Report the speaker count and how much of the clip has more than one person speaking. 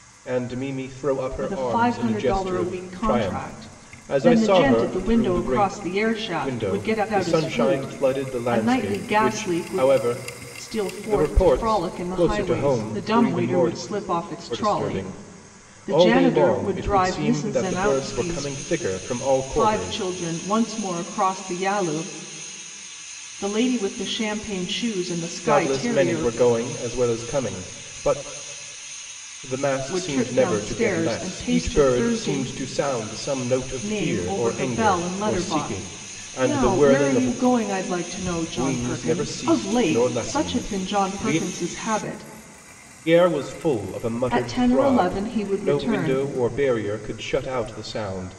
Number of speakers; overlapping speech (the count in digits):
2, about 52%